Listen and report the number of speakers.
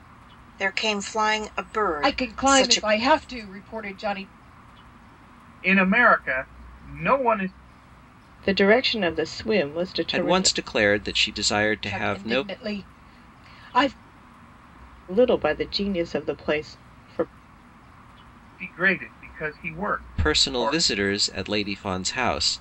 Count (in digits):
5